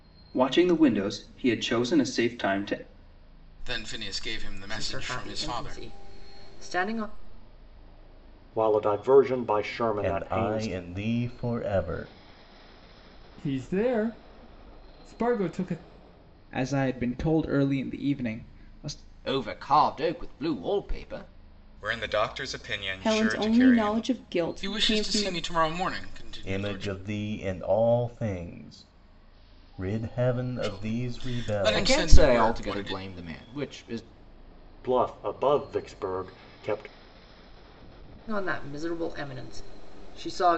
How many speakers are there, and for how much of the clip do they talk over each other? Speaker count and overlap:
ten, about 17%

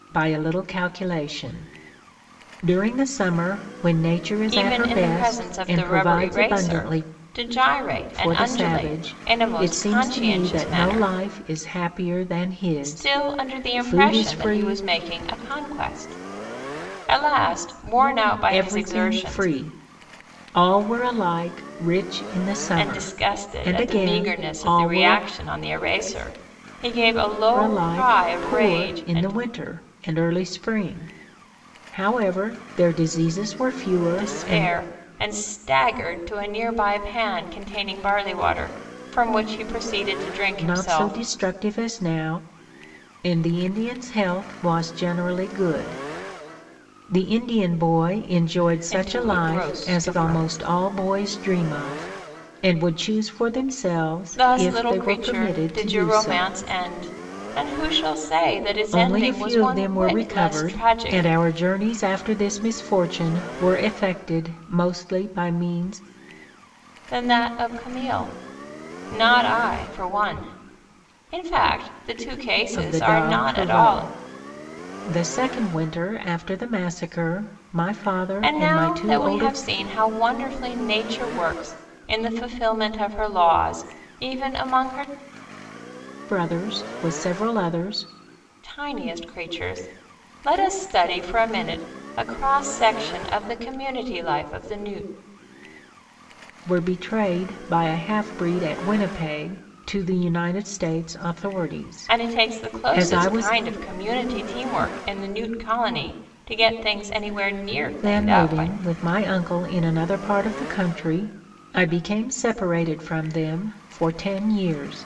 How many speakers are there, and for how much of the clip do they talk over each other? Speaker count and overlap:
two, about 22%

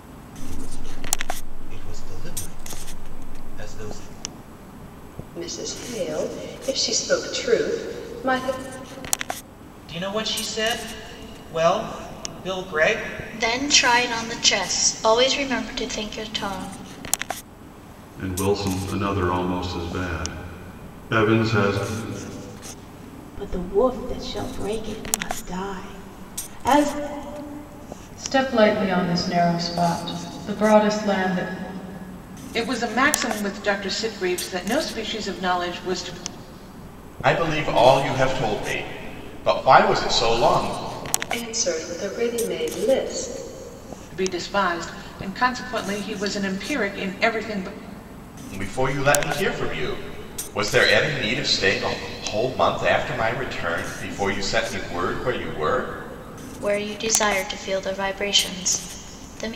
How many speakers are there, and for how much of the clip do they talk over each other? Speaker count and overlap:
nine, no overlap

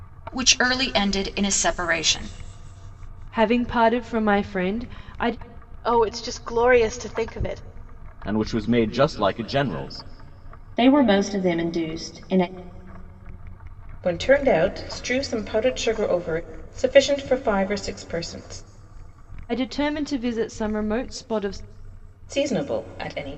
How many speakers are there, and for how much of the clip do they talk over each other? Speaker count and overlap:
six, no overlap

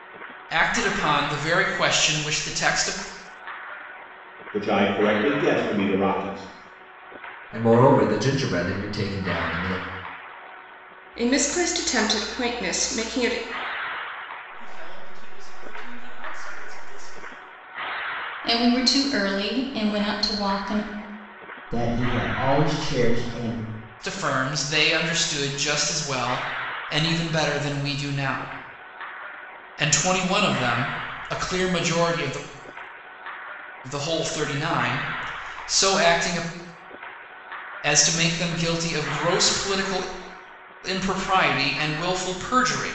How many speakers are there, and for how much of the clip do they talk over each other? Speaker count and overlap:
seven, no overlap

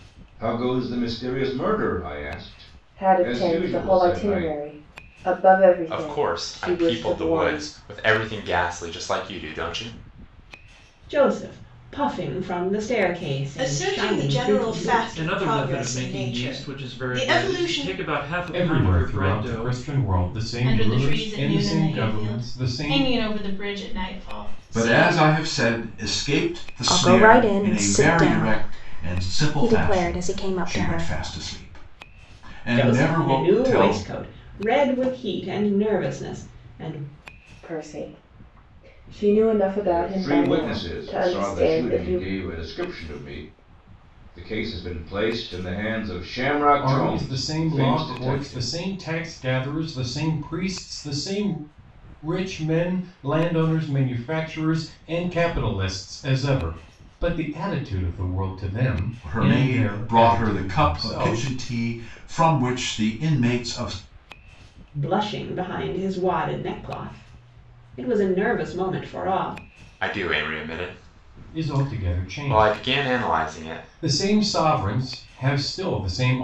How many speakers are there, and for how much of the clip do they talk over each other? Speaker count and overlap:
ten, about 35%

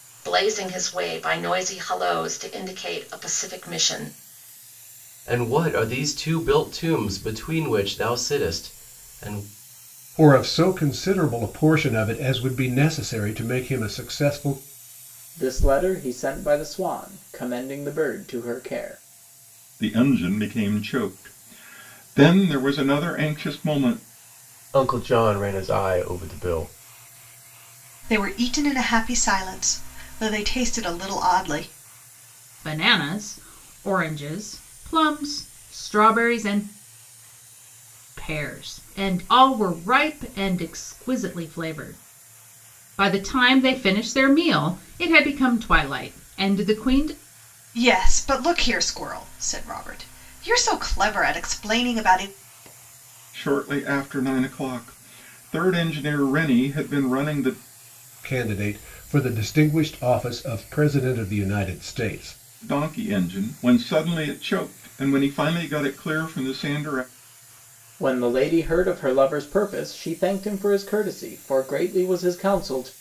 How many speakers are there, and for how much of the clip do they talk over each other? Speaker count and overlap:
eight, no overlap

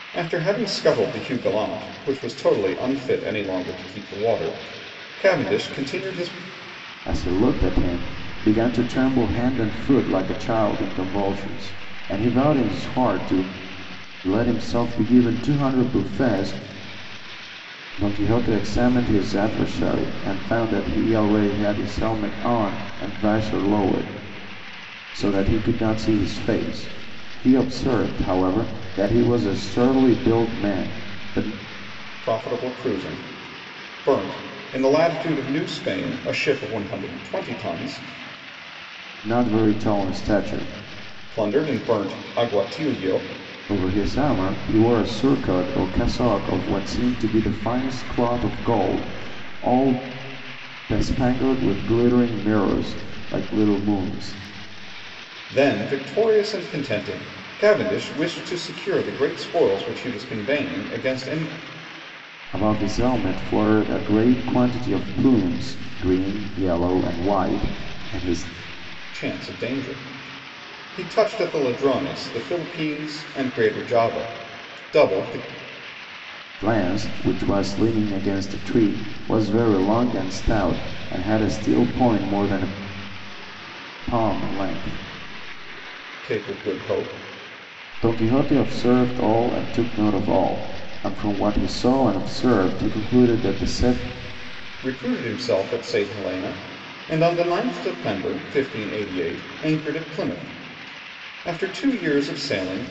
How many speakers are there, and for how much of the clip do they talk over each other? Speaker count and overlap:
two, no overlap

